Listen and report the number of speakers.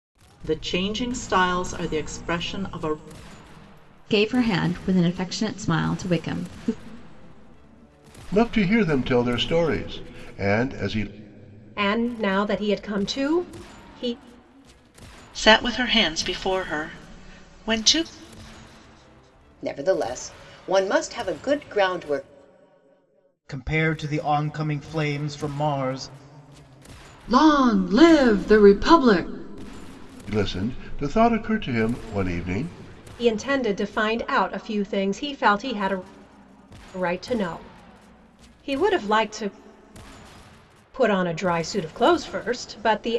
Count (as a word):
eight